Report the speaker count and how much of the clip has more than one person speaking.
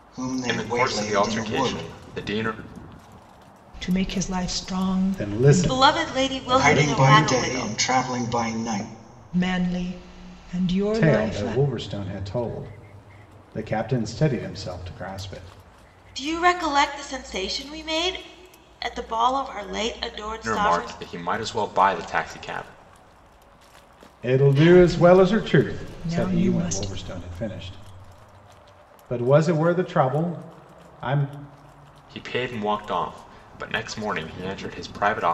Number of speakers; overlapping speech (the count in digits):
5, about 21%